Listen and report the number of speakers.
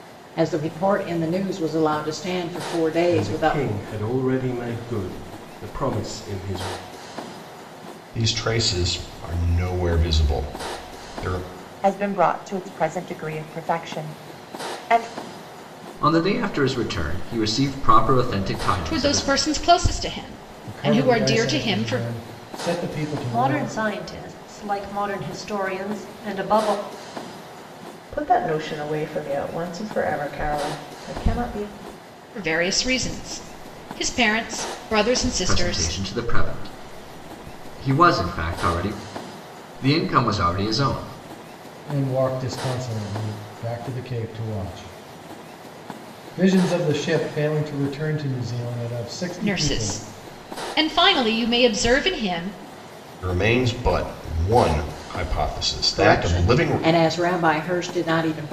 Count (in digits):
9